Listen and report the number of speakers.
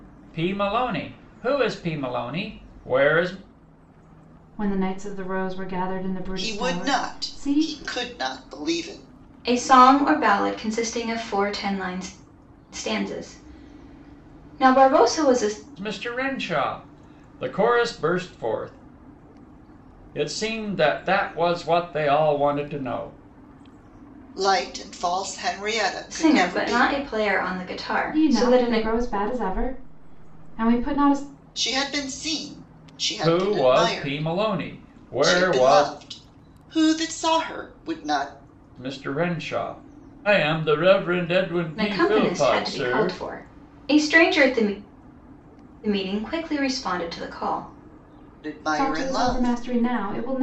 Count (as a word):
four